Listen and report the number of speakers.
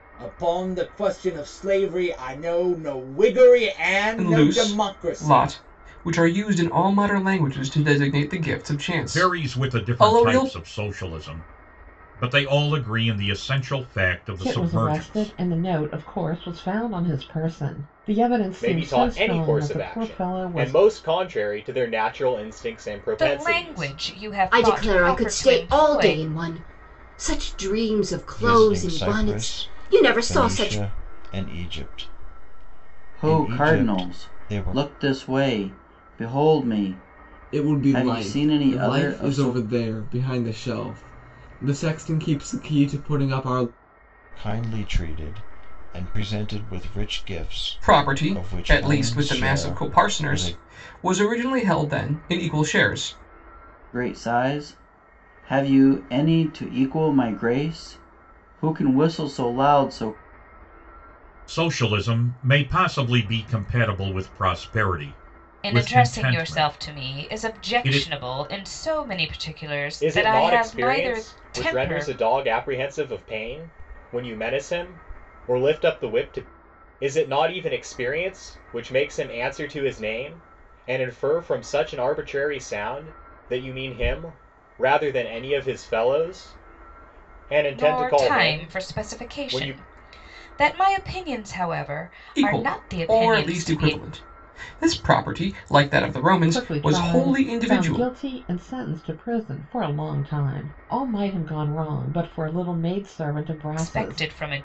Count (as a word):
ten